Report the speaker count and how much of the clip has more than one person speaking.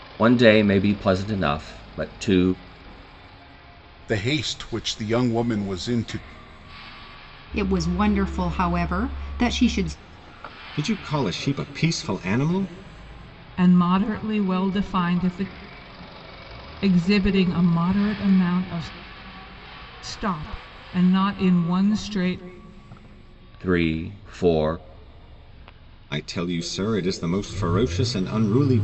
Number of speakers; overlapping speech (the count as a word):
five, no overlap